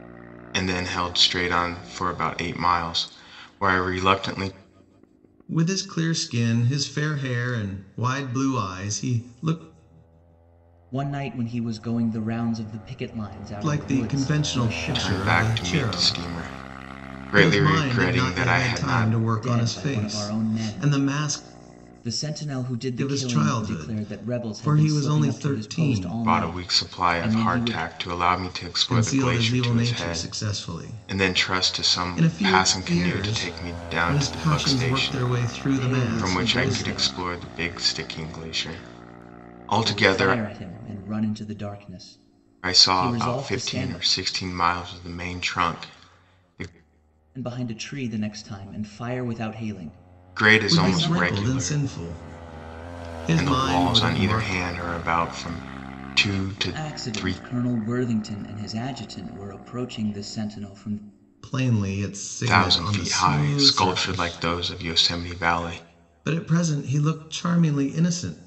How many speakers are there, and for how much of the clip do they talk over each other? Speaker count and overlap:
3, about 38%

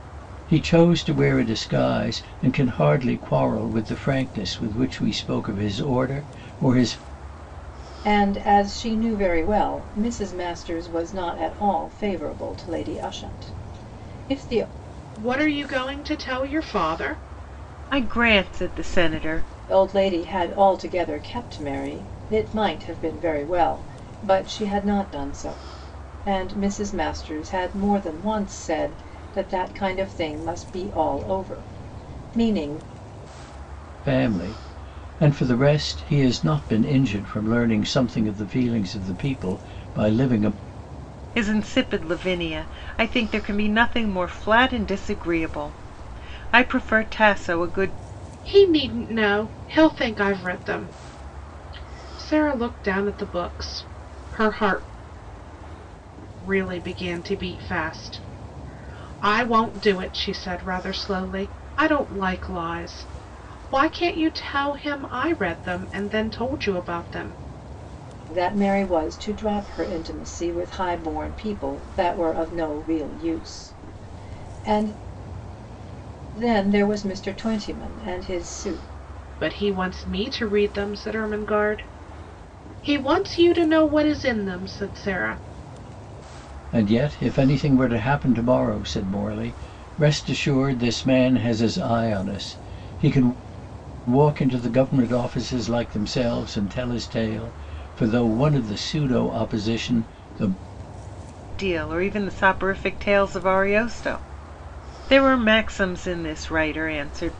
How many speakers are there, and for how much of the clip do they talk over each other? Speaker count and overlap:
4, no overlap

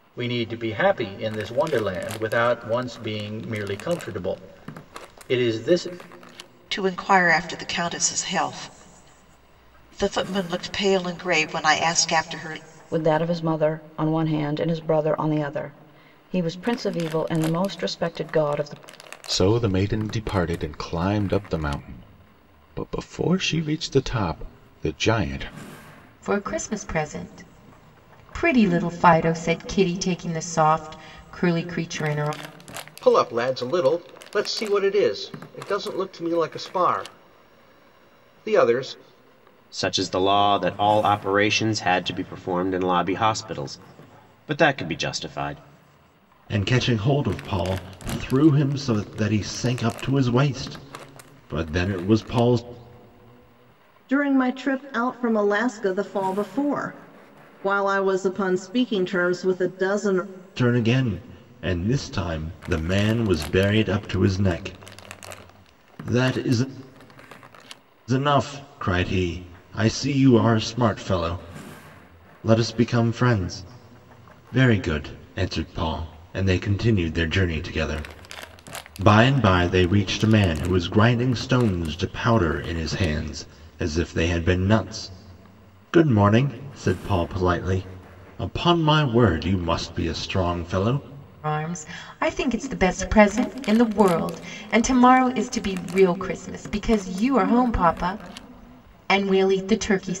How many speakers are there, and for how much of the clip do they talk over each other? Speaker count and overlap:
9, no overlap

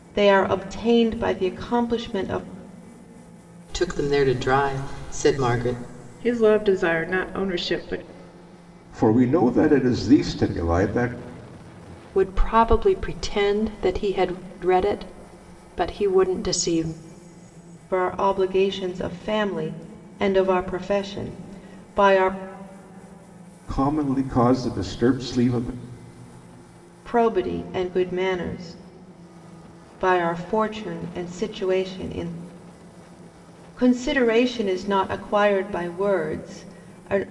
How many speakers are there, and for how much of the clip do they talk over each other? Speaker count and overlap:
5, no overlap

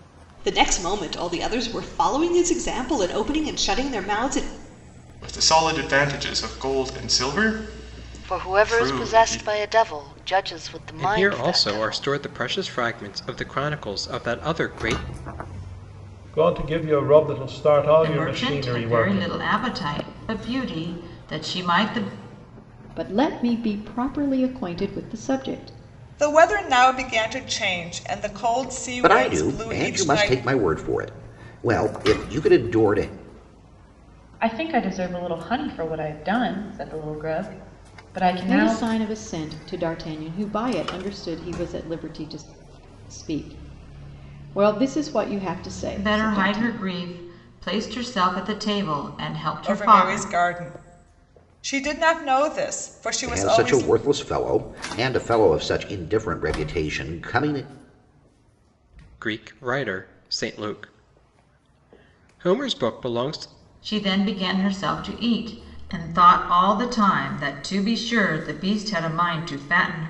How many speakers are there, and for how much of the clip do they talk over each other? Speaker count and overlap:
10, about 11%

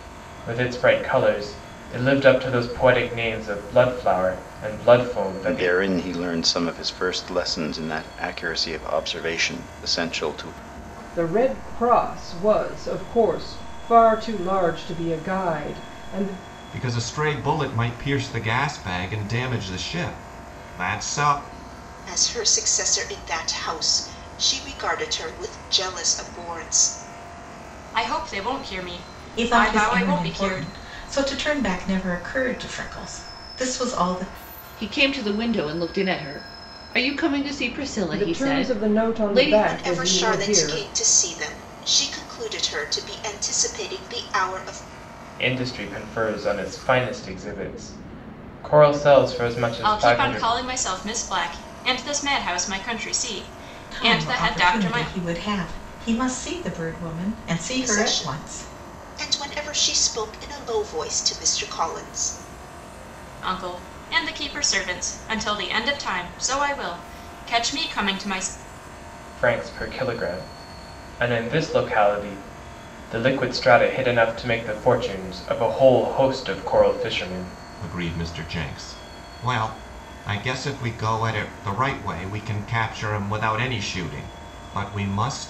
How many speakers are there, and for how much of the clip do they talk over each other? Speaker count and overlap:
8, about 9%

